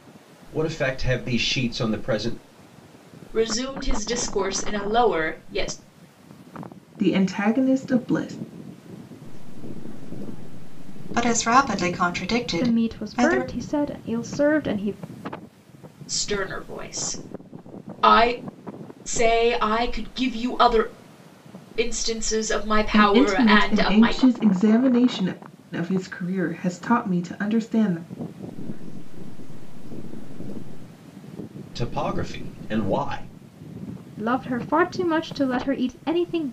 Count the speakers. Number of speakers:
six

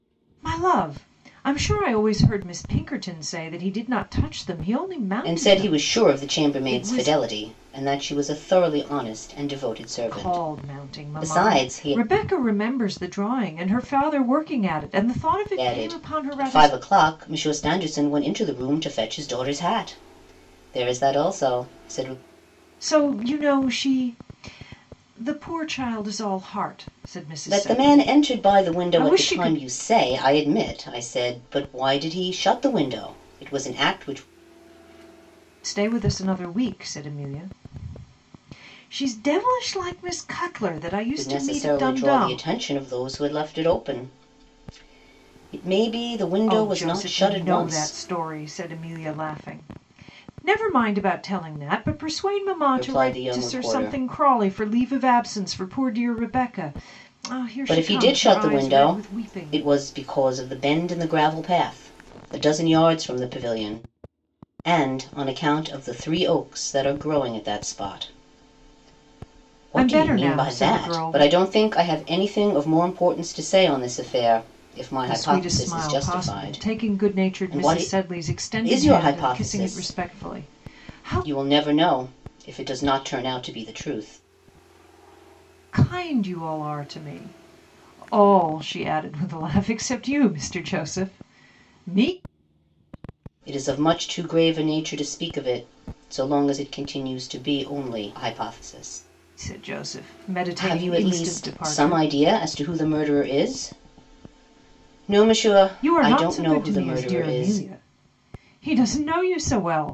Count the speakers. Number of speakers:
two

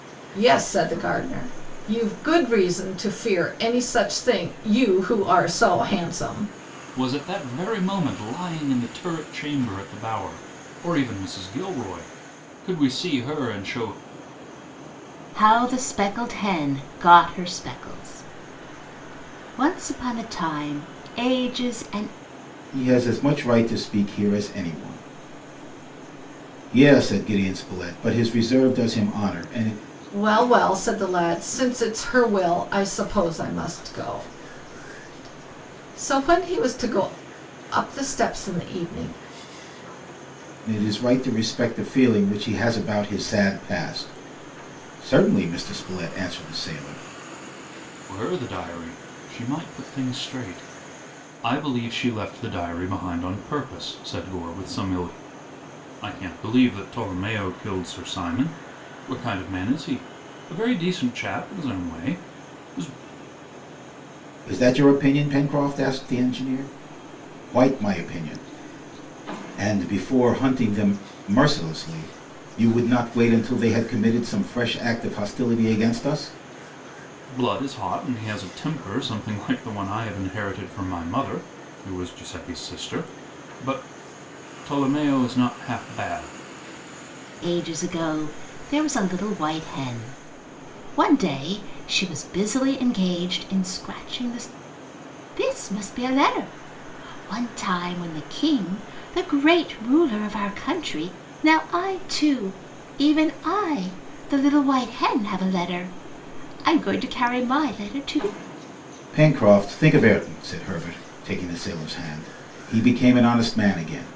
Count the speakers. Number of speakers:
four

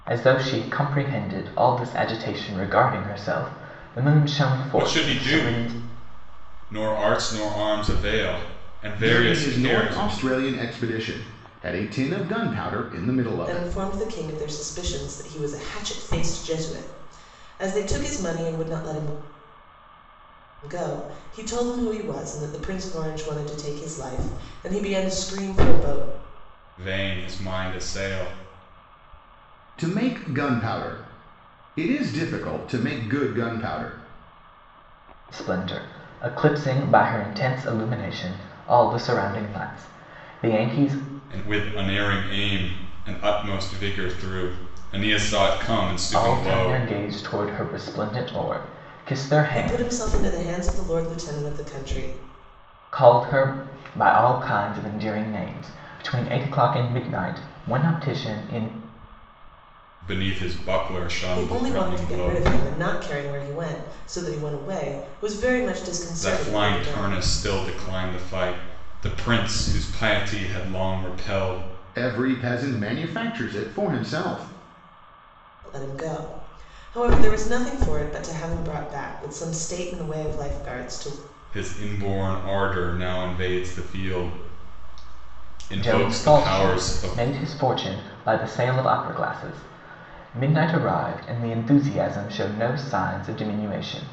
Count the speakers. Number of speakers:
four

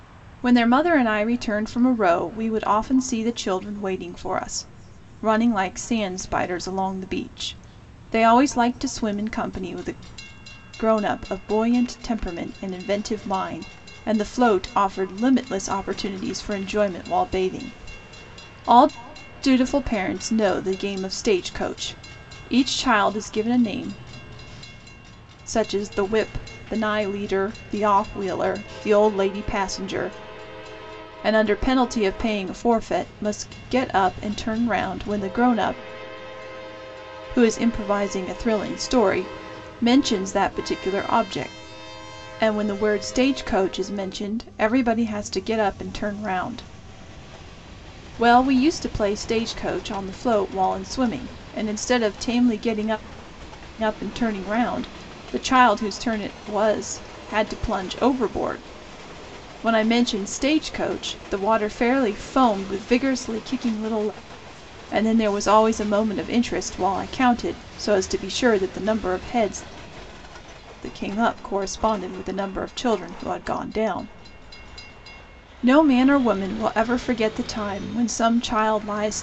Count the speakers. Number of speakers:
one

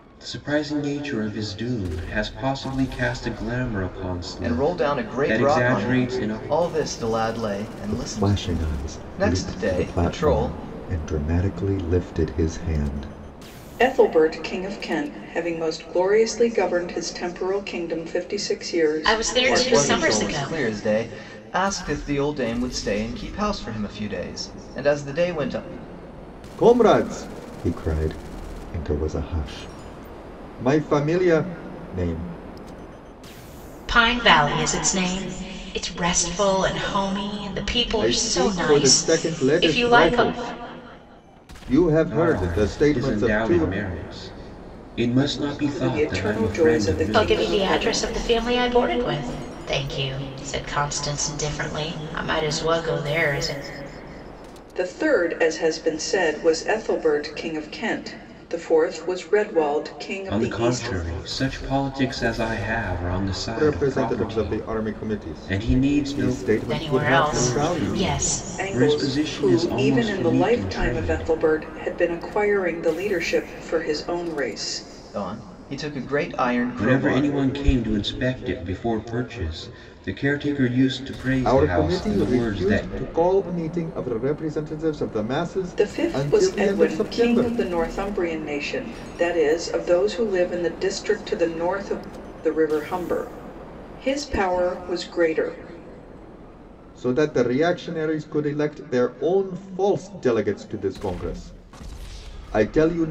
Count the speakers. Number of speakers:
five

